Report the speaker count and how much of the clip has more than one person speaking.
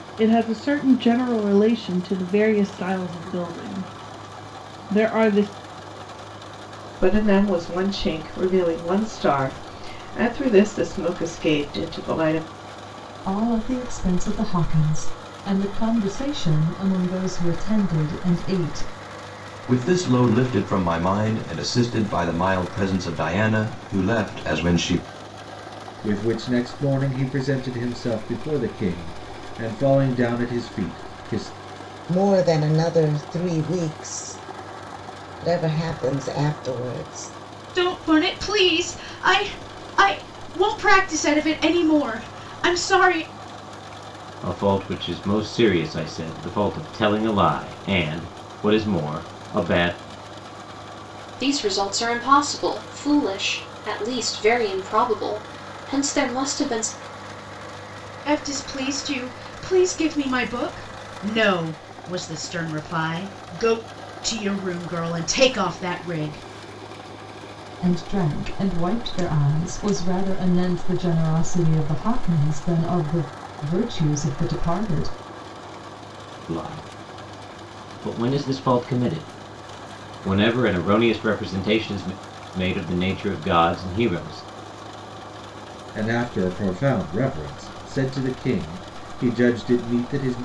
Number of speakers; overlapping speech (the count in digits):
9, no overlap